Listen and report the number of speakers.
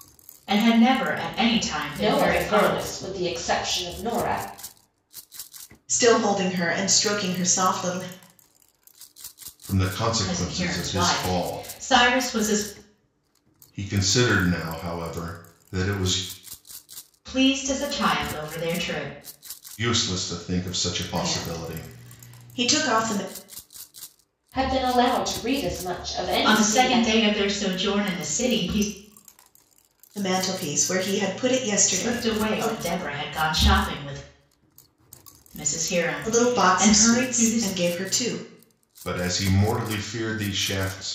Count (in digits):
4